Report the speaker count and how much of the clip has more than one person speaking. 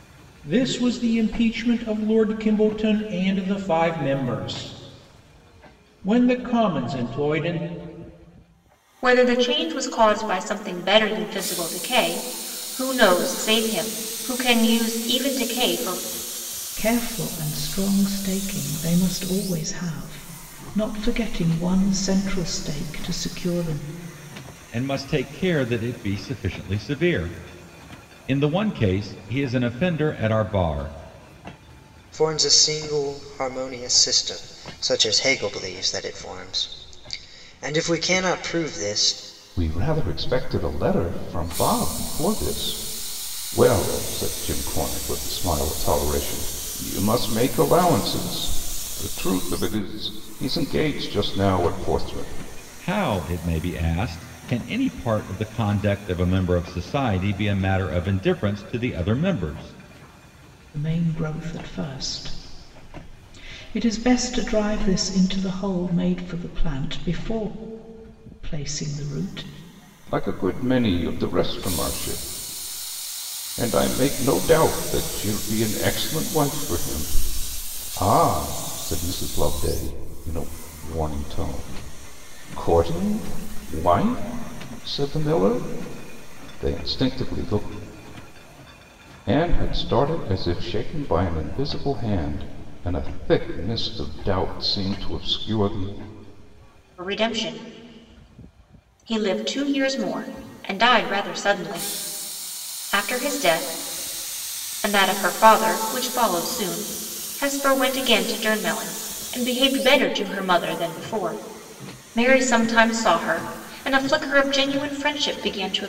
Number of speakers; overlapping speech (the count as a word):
six, no overlap